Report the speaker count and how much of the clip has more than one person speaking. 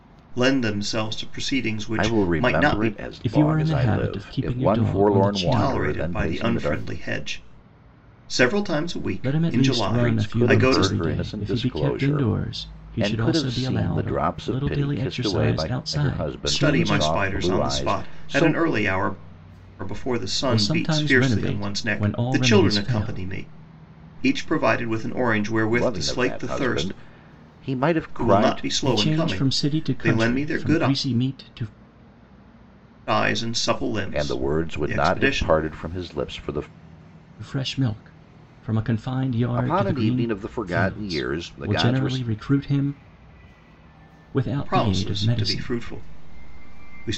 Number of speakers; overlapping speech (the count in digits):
3, about 52%